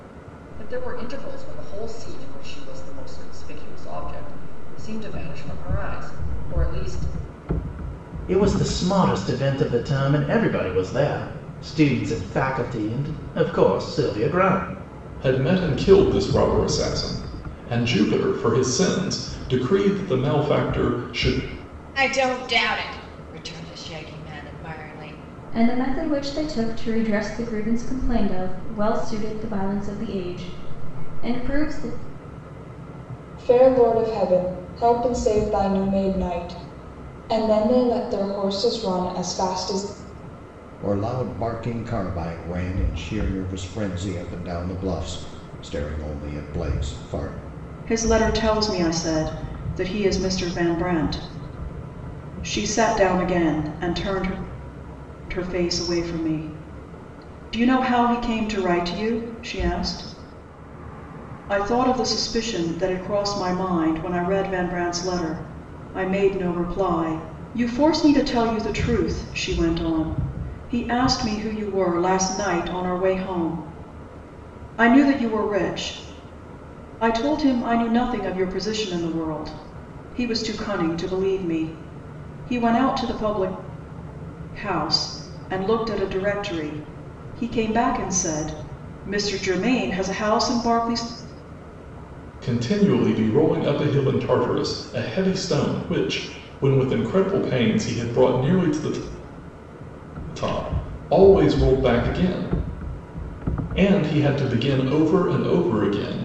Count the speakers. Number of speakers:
eight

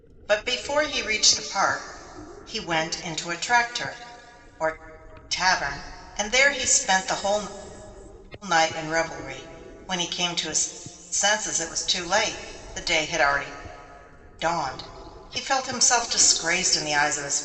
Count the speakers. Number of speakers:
one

